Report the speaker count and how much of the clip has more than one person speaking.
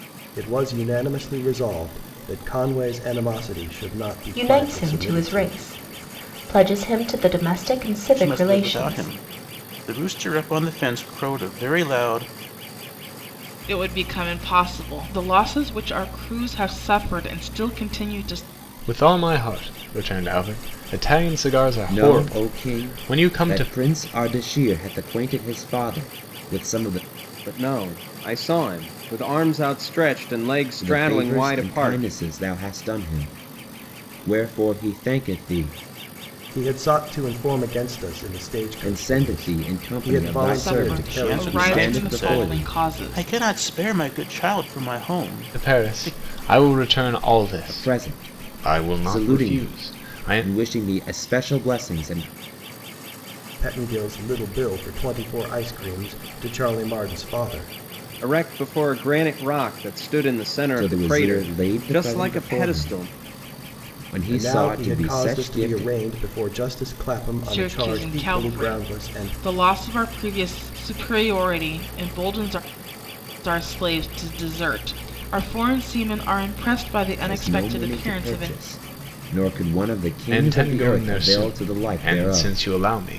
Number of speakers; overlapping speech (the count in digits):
7, about 28%